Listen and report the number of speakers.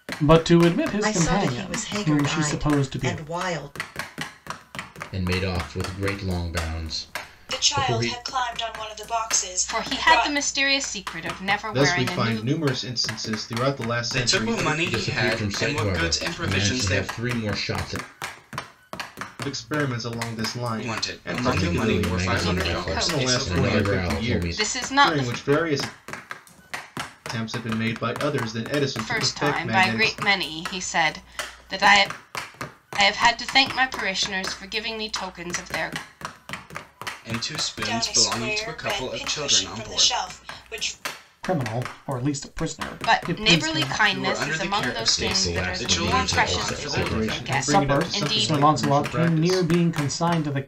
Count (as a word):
seven